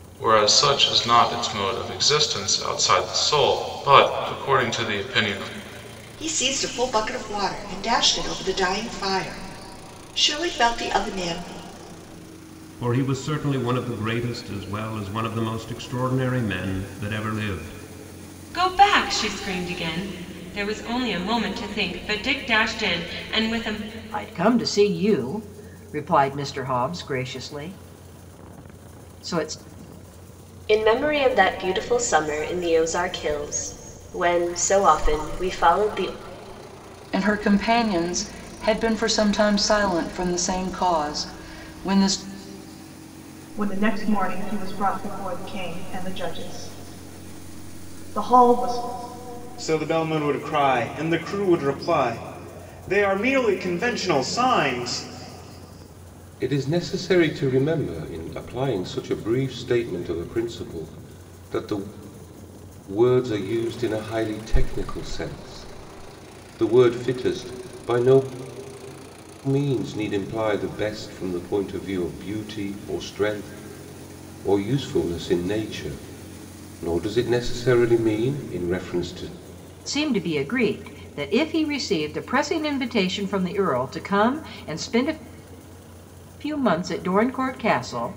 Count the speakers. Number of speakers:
ten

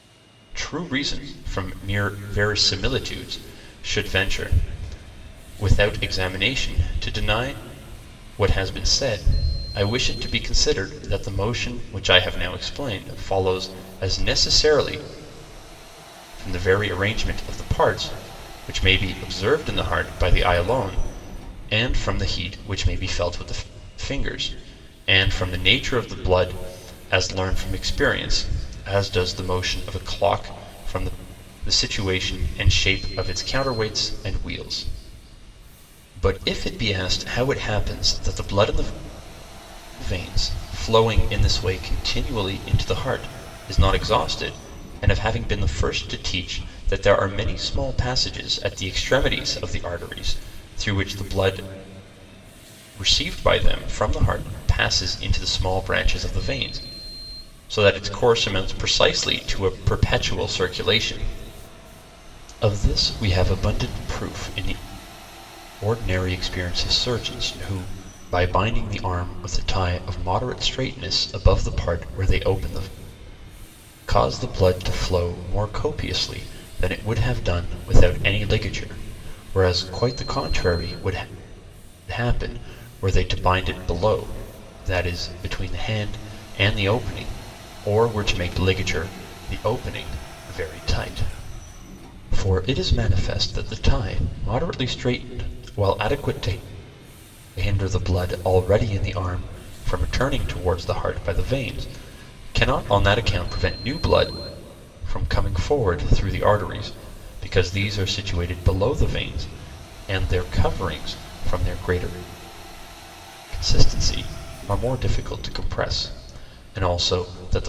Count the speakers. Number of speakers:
one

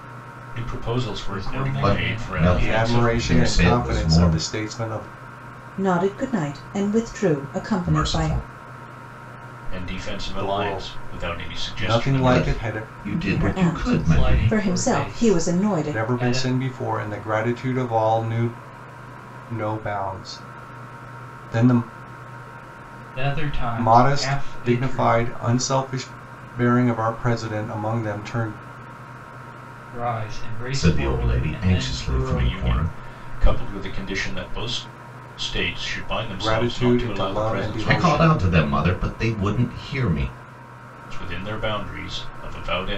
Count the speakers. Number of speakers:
five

